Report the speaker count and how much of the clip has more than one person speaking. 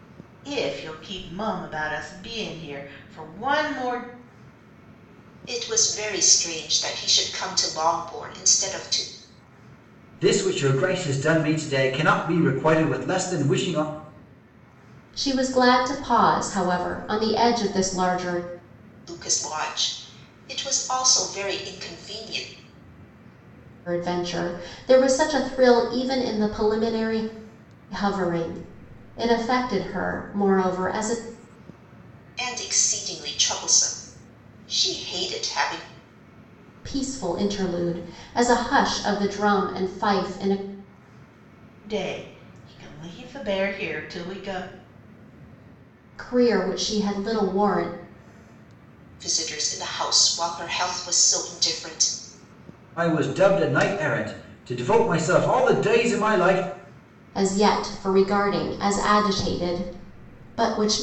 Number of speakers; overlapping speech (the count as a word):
four, no overlap